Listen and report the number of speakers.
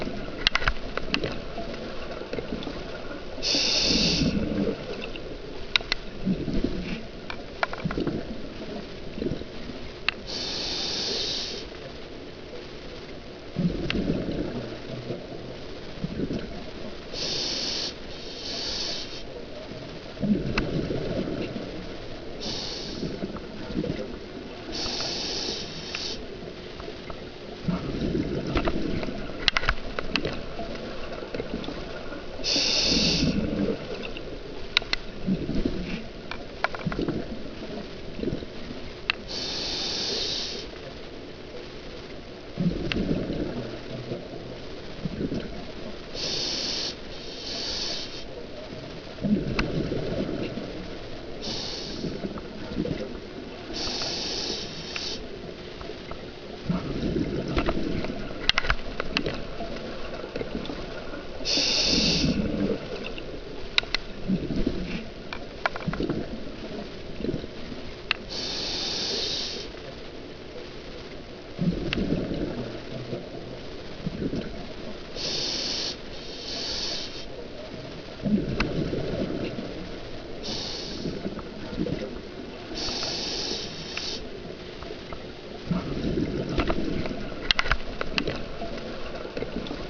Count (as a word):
zero